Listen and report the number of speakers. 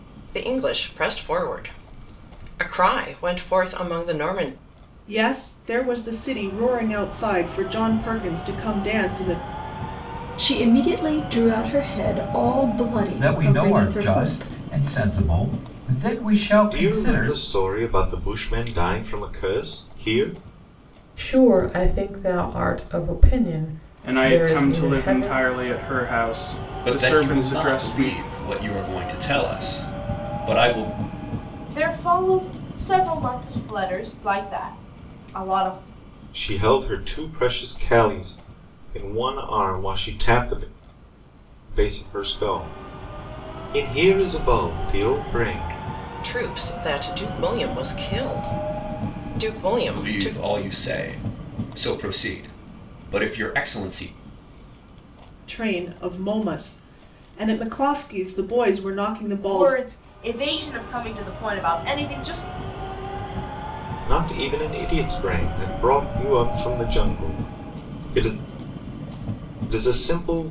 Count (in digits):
9